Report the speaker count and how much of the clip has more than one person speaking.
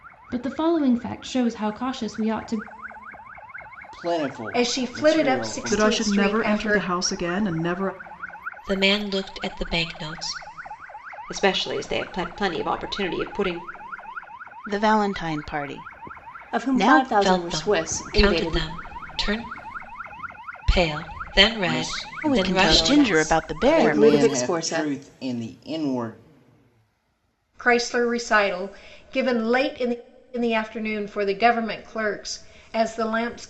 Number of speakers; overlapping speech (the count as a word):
eight, about 23%